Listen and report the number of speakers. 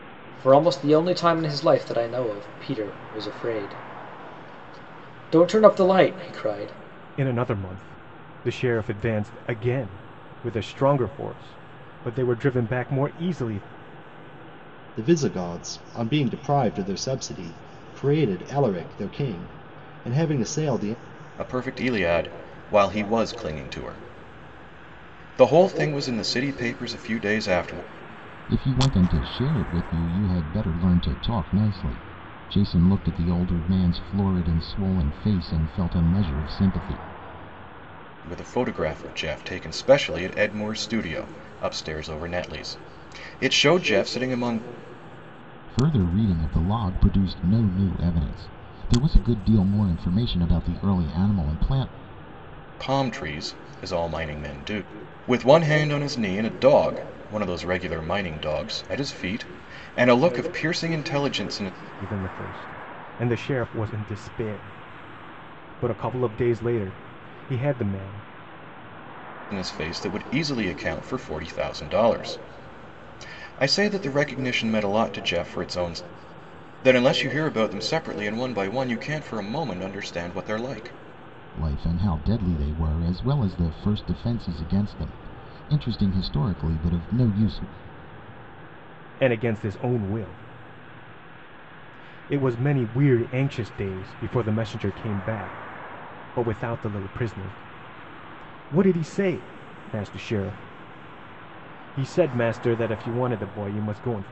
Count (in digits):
5